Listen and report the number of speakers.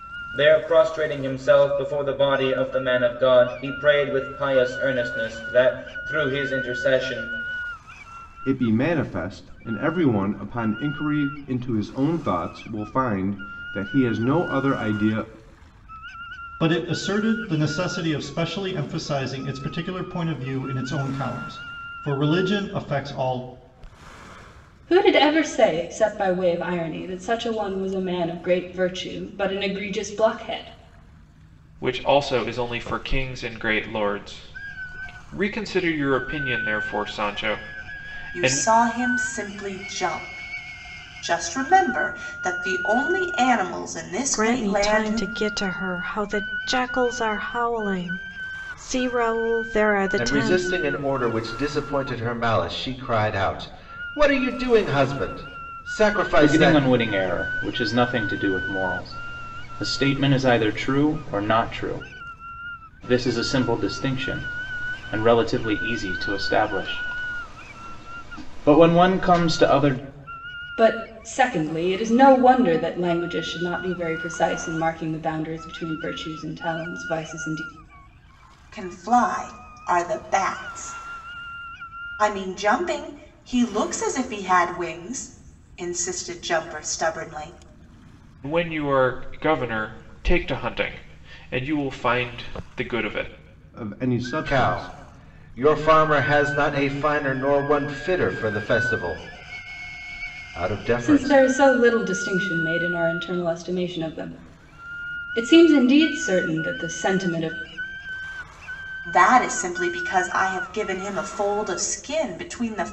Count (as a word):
nine